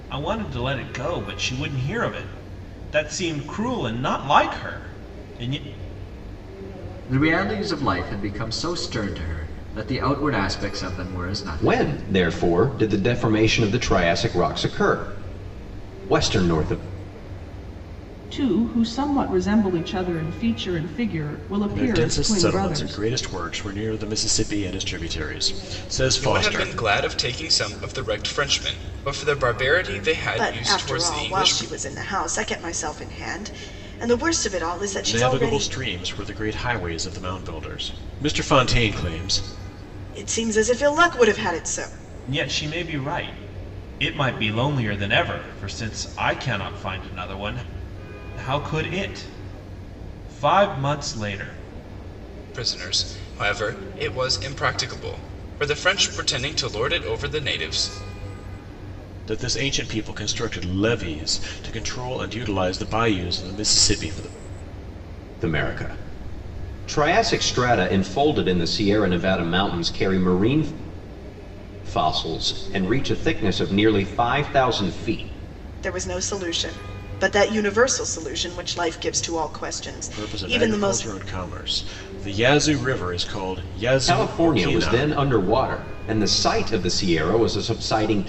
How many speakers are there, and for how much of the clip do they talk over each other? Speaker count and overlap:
7, about 7%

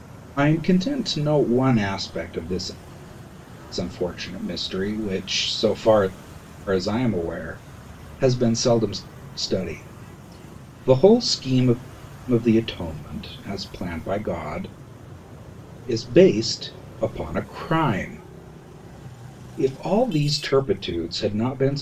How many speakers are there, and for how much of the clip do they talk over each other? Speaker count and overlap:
1, no overlap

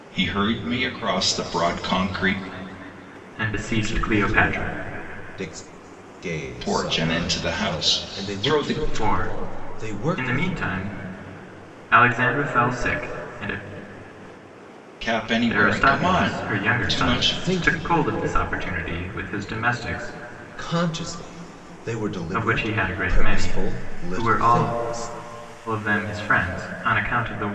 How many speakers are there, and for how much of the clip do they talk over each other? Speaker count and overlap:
3, about 36%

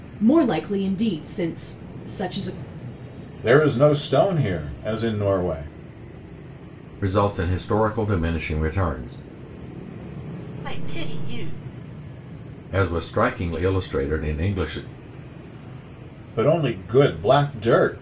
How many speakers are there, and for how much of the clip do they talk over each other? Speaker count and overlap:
4, no overlap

